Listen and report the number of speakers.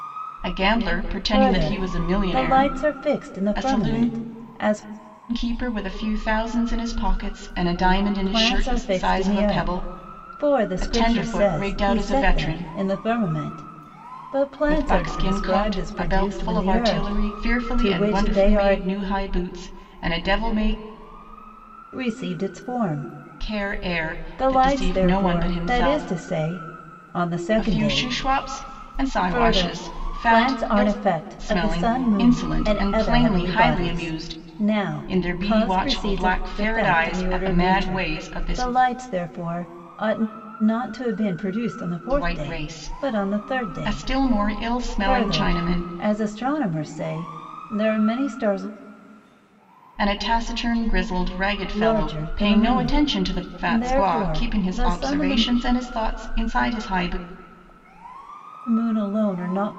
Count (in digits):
2